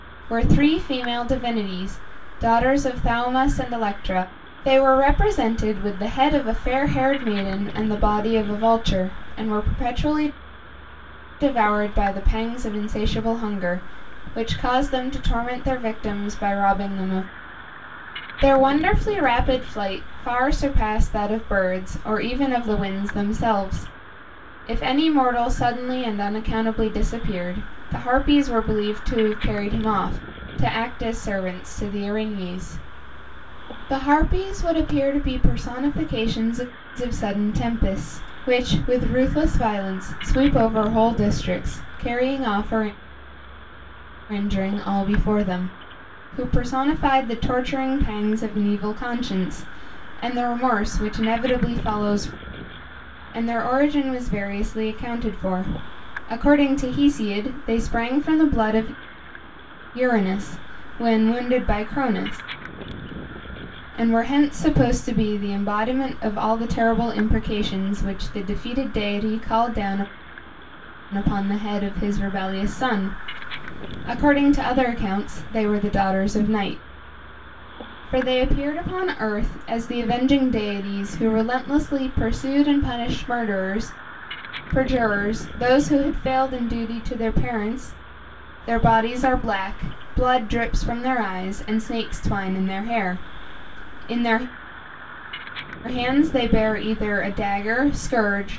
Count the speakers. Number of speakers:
one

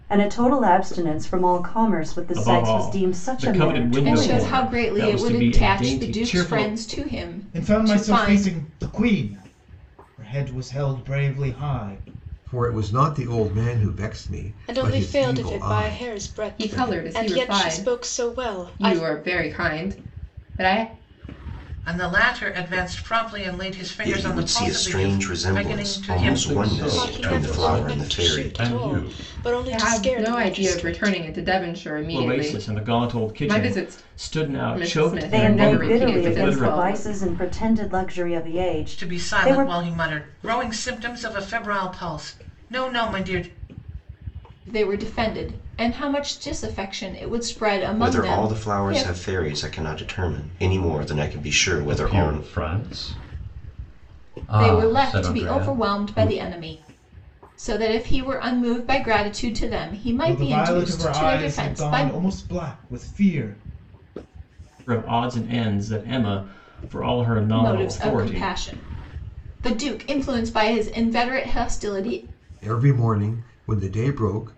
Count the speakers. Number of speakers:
ten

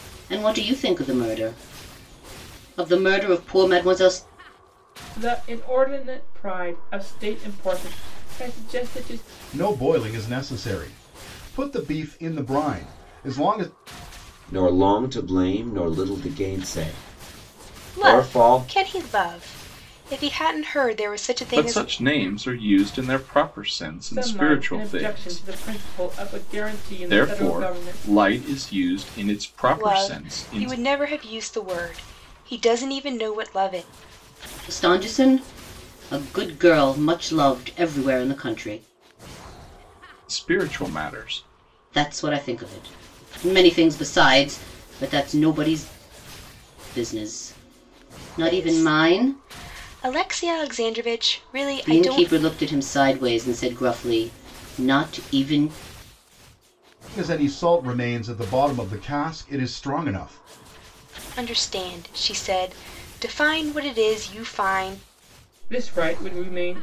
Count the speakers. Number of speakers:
six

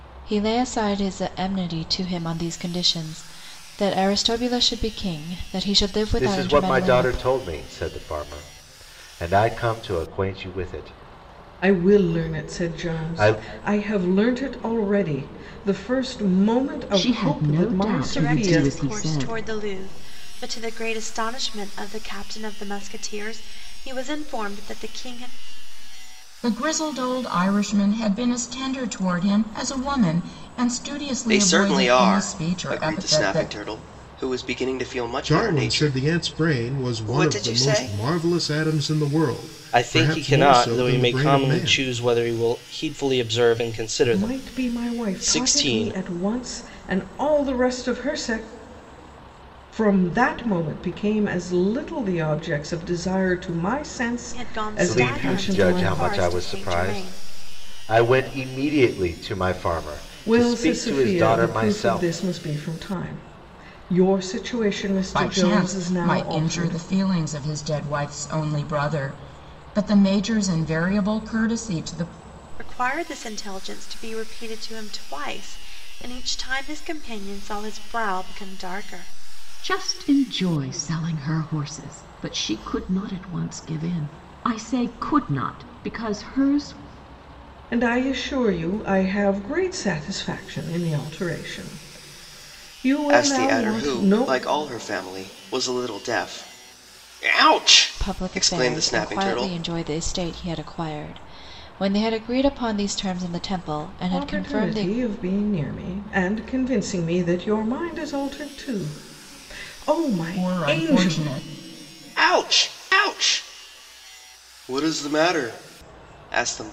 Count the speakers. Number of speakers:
nine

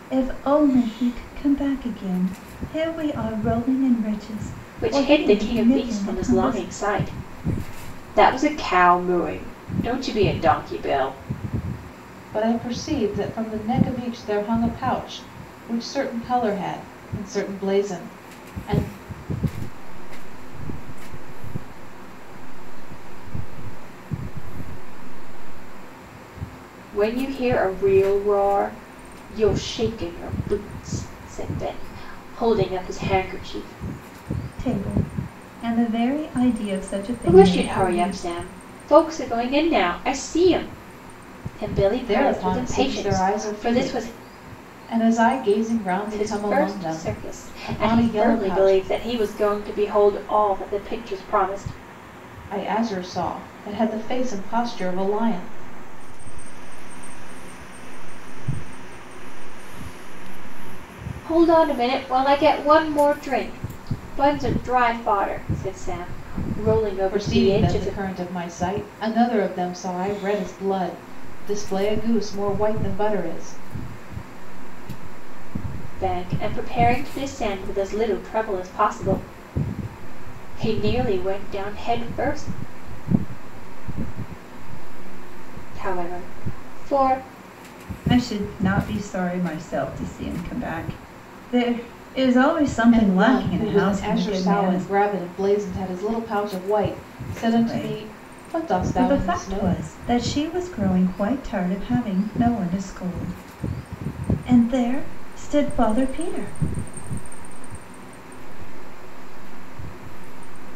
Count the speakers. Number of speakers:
four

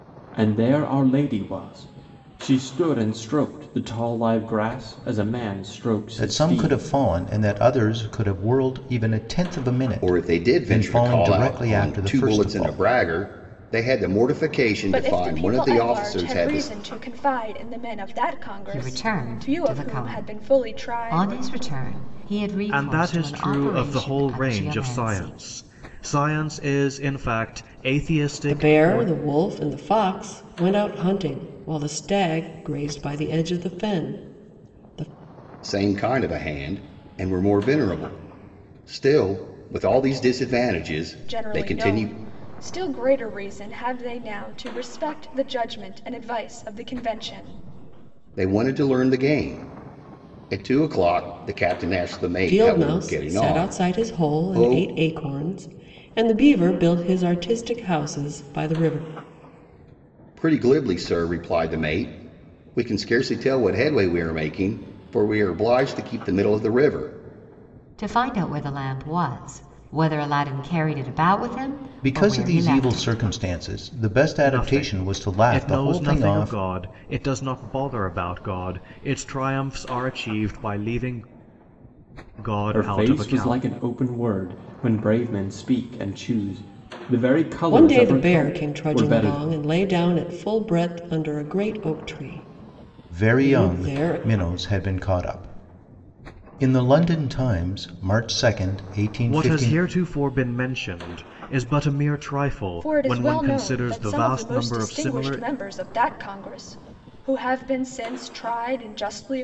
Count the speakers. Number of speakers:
seven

